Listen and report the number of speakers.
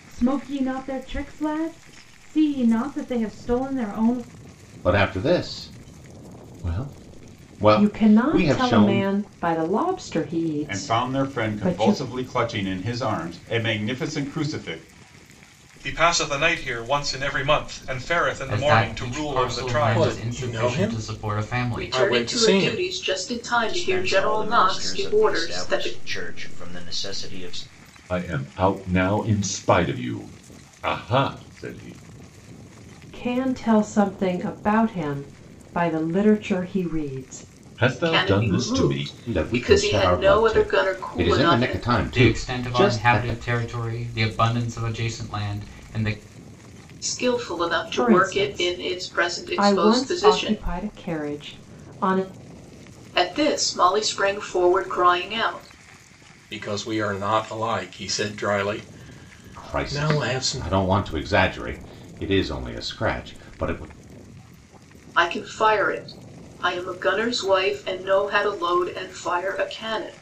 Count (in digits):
10